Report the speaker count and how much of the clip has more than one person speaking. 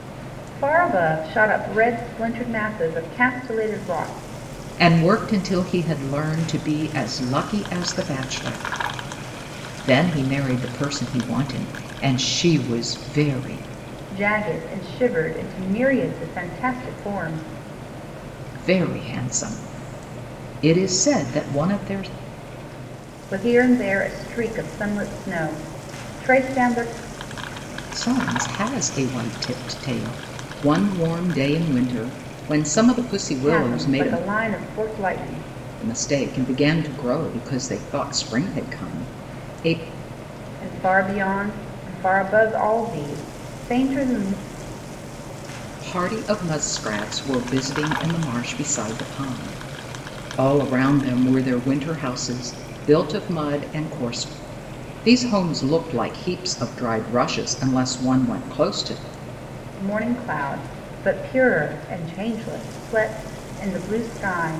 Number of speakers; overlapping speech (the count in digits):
2, about 1%